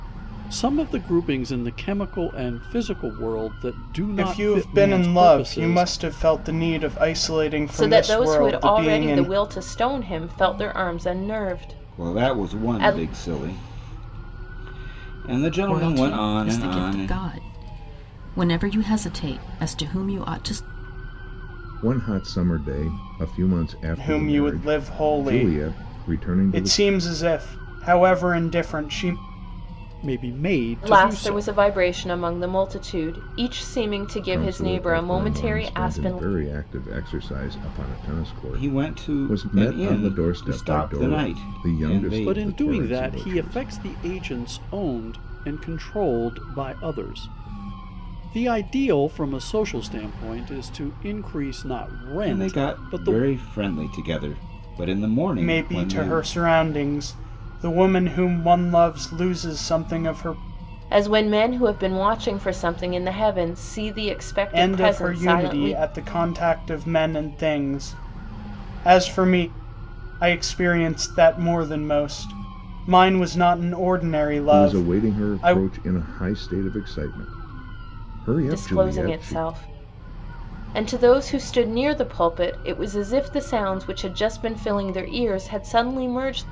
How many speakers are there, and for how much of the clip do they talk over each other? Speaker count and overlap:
6, about 26%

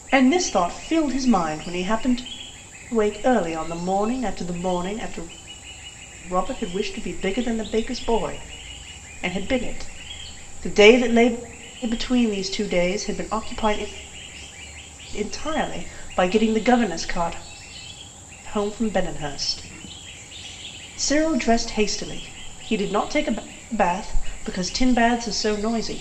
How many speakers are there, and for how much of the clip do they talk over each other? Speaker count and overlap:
1, no overlap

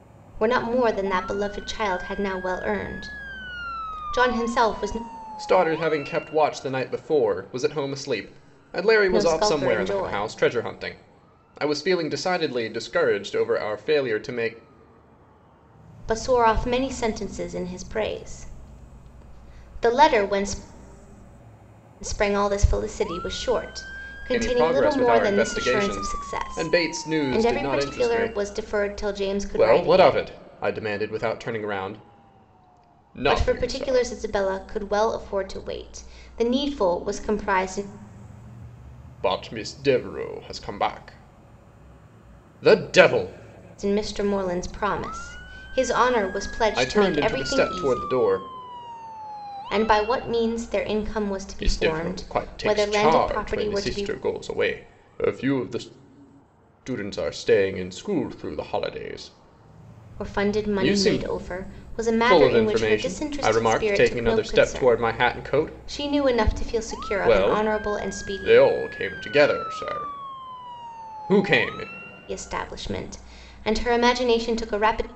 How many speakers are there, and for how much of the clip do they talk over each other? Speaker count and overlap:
2, about 22%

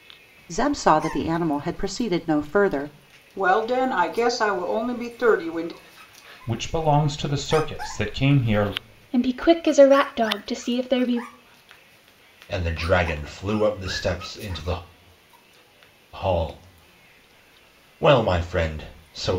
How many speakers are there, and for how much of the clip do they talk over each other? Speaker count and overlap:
5, no overlap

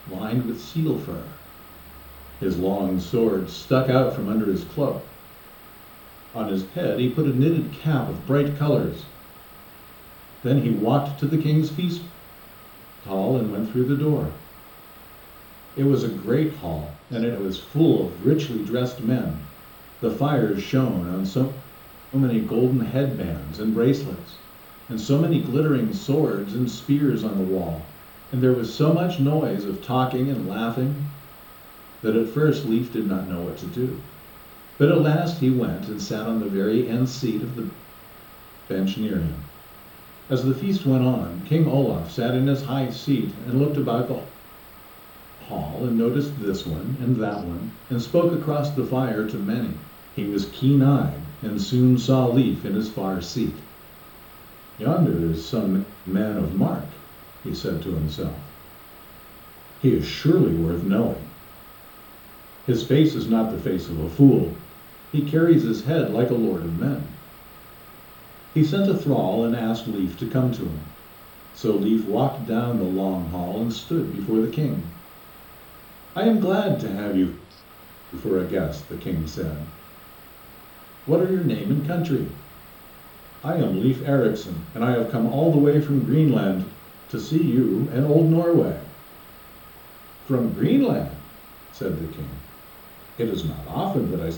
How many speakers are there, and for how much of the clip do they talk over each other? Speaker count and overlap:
1, no overlap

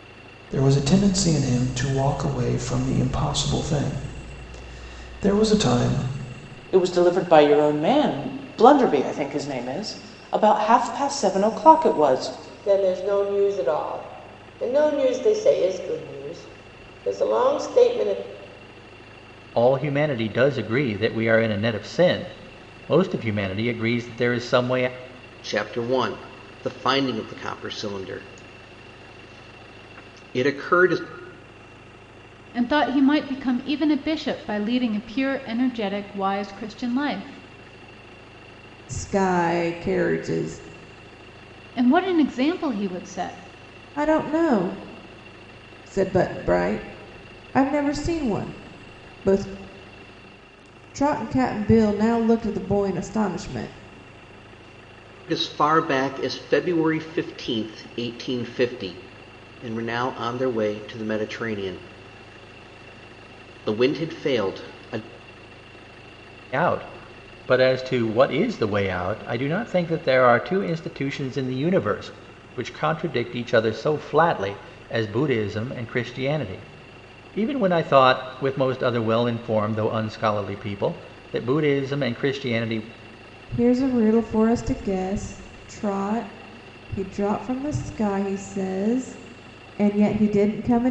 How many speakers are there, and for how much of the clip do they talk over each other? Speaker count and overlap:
7, no overlap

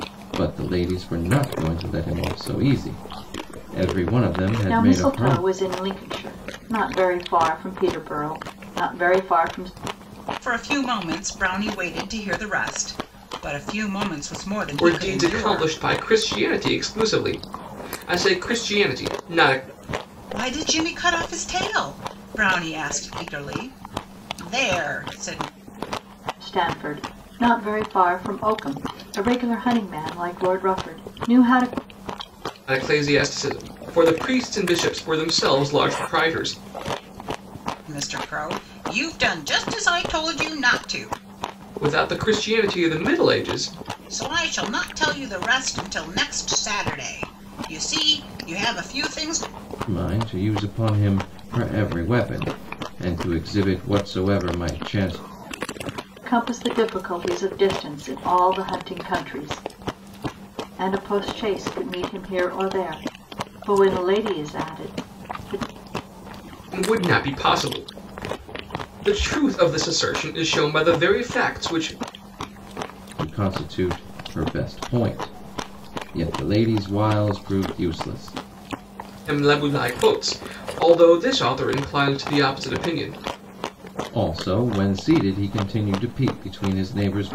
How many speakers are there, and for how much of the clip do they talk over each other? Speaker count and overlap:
4, about 2%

